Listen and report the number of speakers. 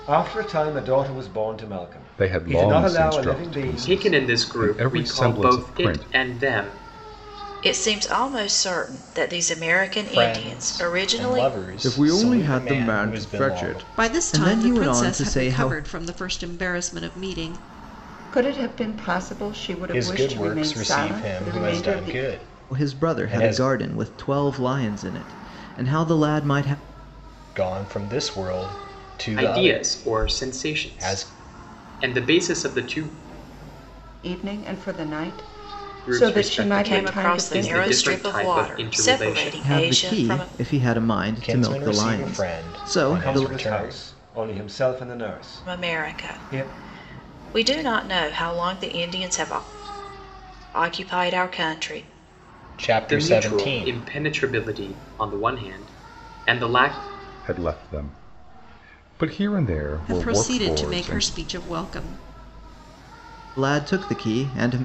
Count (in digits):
8